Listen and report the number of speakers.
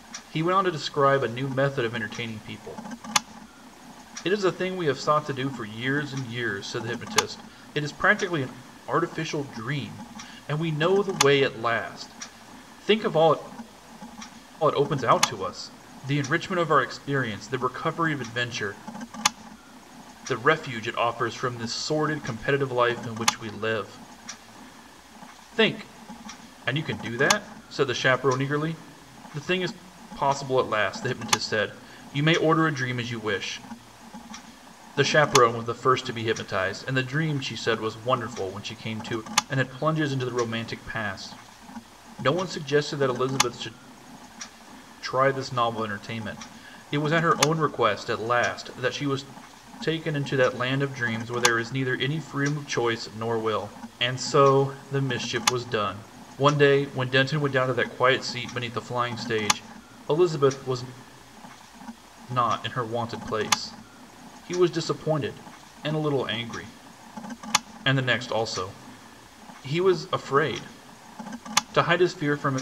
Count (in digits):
1